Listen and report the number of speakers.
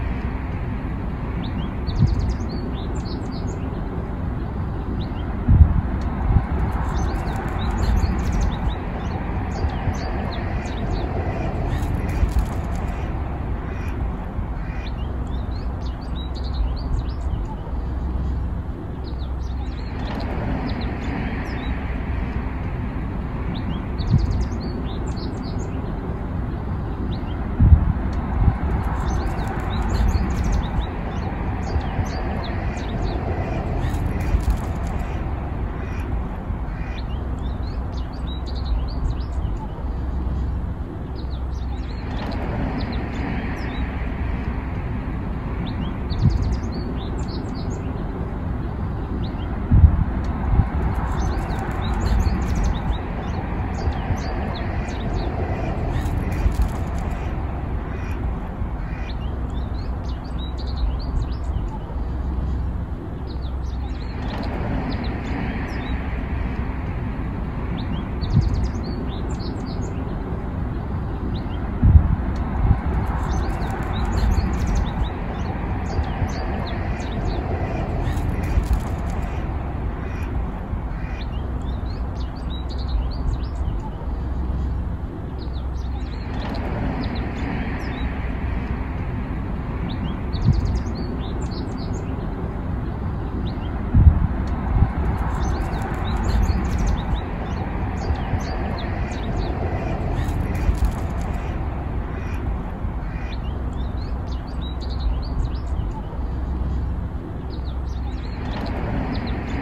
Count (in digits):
0